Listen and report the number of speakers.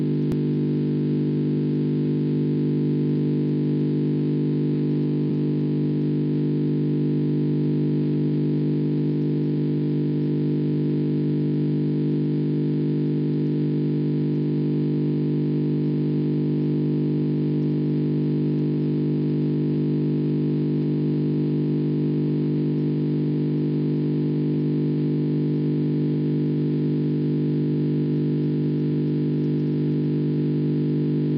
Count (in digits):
0